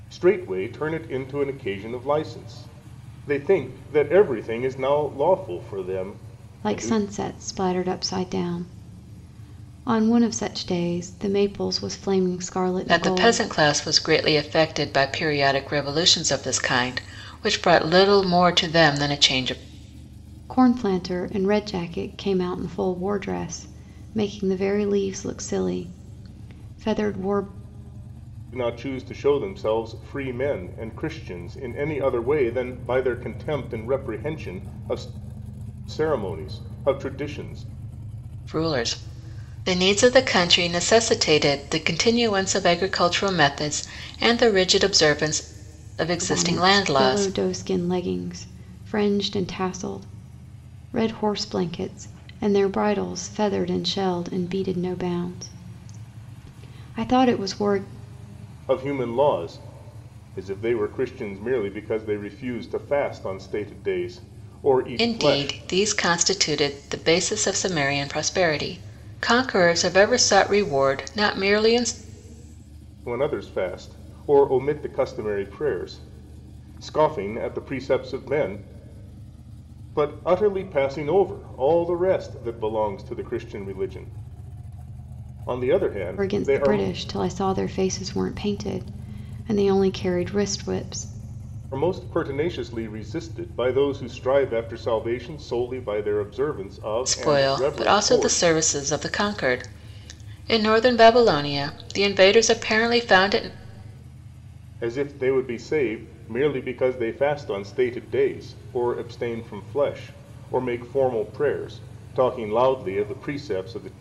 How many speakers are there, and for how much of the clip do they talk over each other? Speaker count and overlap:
3, about 4%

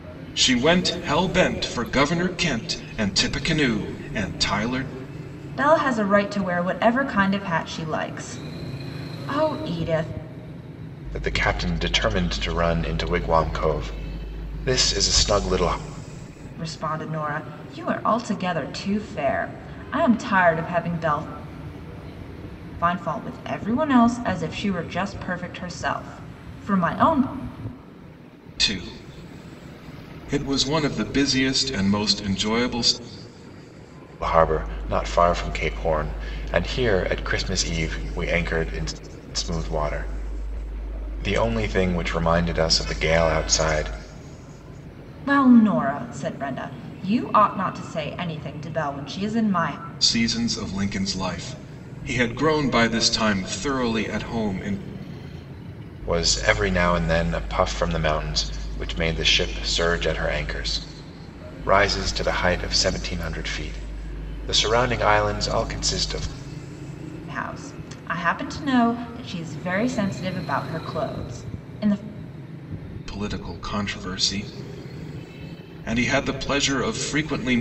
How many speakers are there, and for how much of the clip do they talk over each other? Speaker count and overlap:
3, no overlap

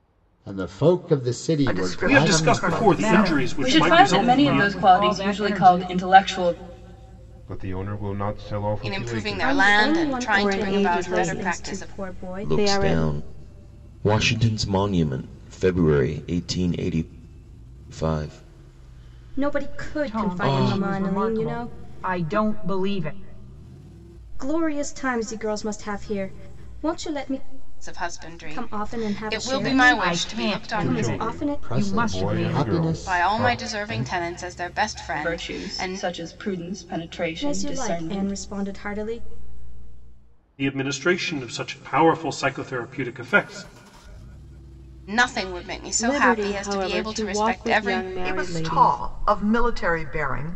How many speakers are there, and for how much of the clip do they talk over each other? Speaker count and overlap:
10, about 44%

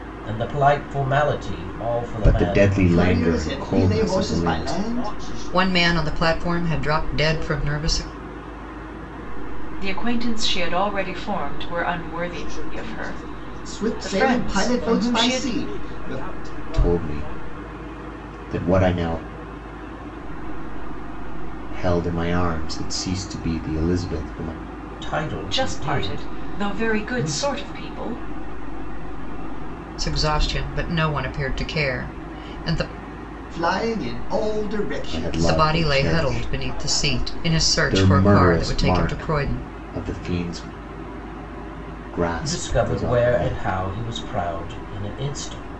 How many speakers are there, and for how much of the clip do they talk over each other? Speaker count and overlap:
8, about 52%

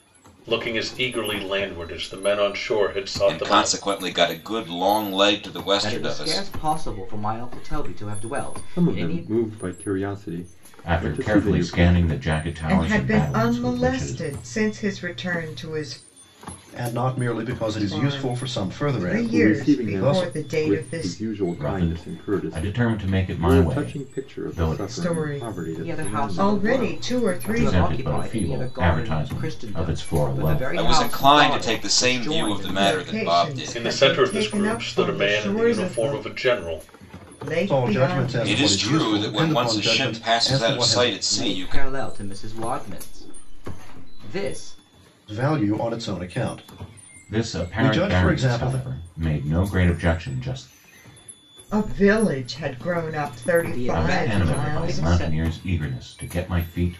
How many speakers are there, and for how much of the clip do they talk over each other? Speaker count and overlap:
7, about 52%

